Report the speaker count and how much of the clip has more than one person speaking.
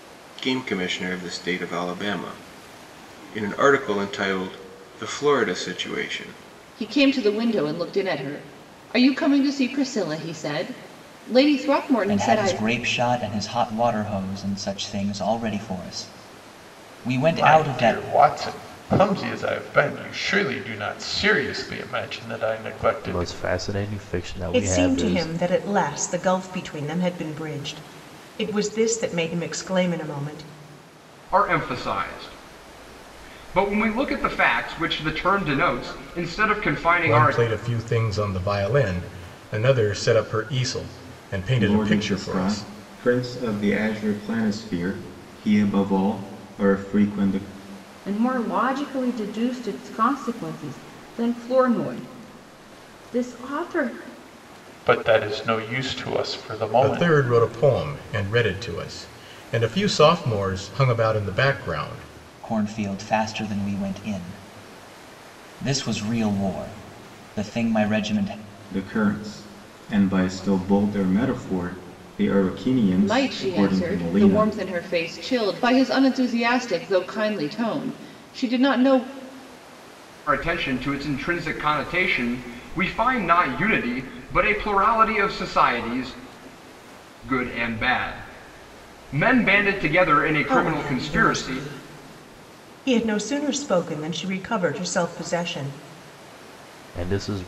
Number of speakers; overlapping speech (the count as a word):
ten, about 7%